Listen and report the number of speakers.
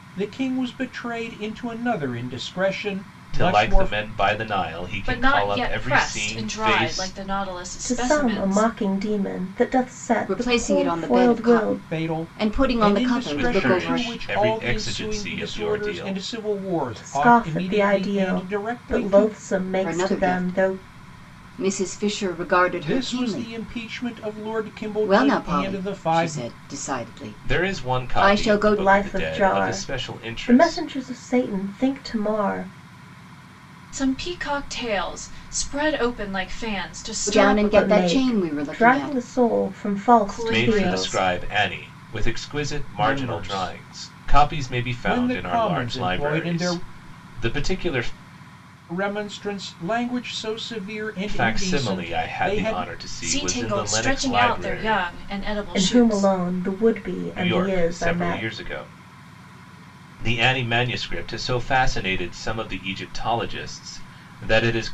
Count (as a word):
five